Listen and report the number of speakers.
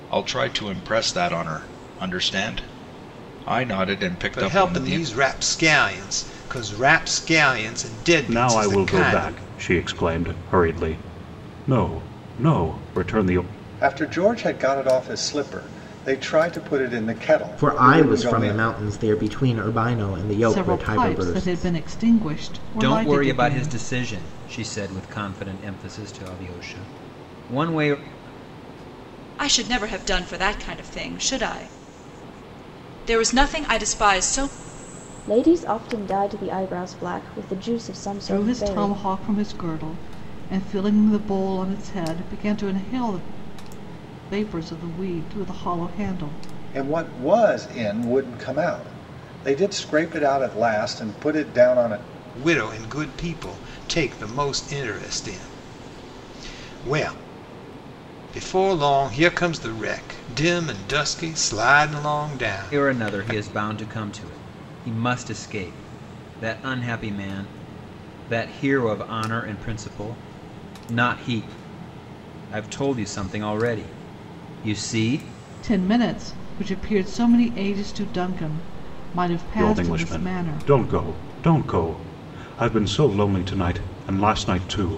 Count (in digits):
9